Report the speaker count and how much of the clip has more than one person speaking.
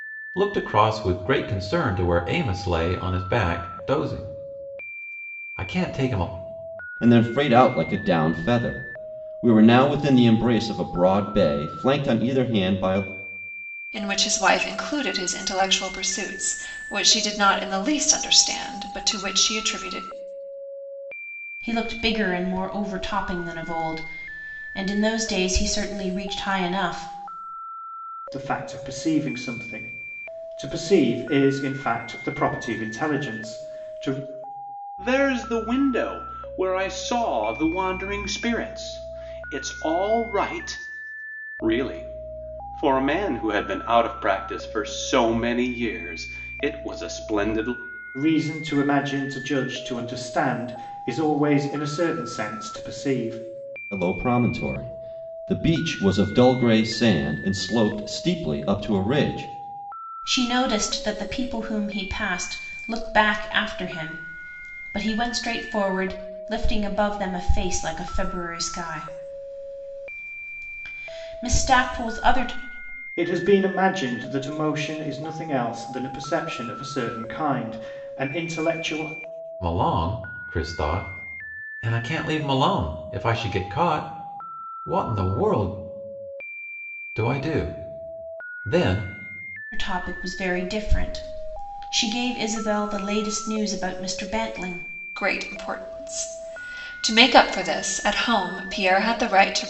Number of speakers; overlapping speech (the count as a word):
six, no overlap